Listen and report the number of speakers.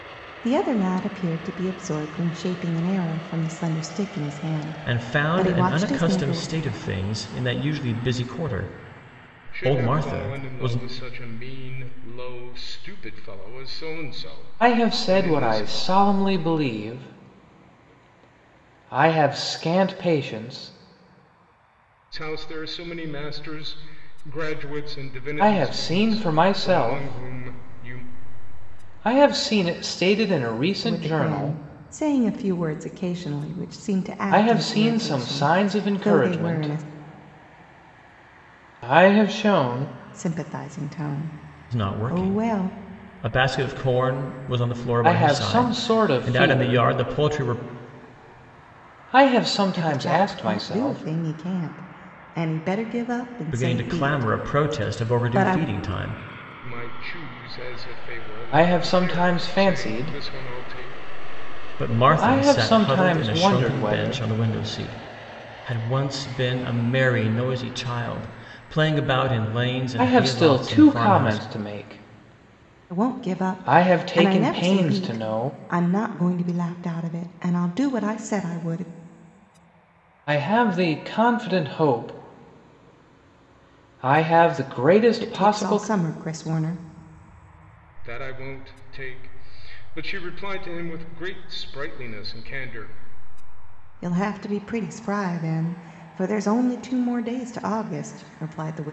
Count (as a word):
four